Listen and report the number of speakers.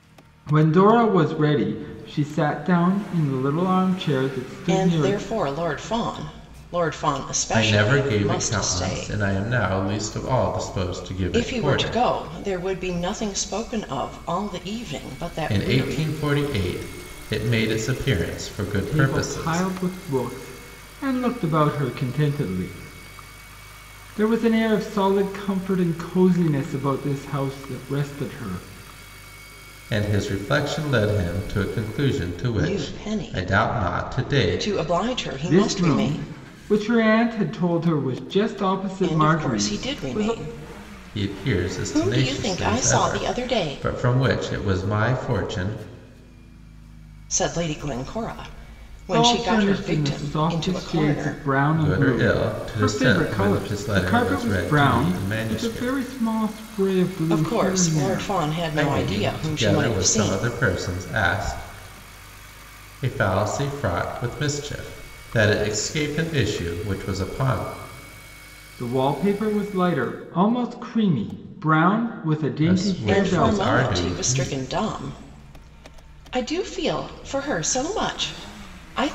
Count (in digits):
3